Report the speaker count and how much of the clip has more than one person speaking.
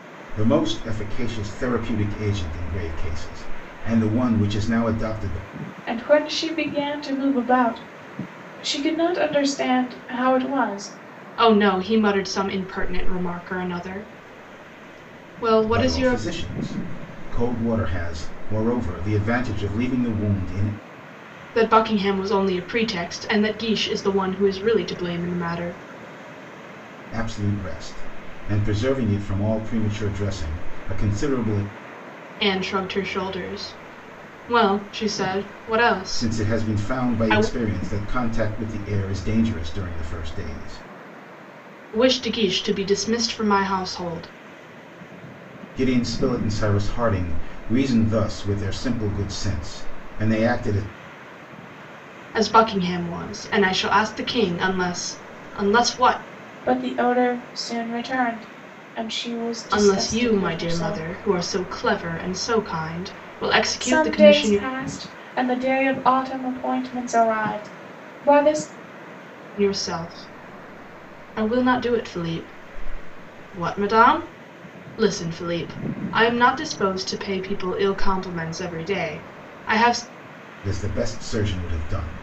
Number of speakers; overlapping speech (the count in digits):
3, about 5%